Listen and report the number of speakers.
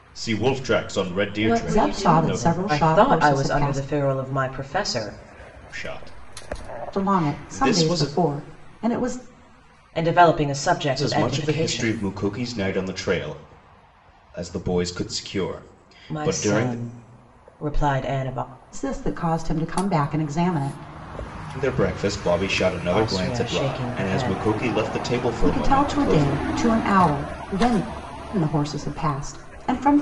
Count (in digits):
3